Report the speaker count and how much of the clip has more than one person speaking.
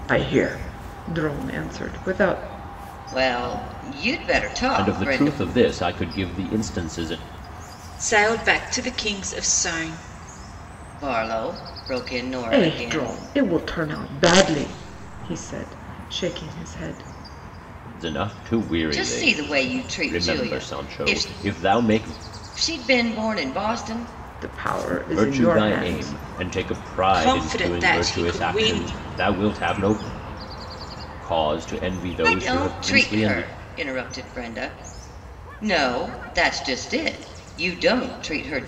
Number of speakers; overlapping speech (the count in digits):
4, about 19%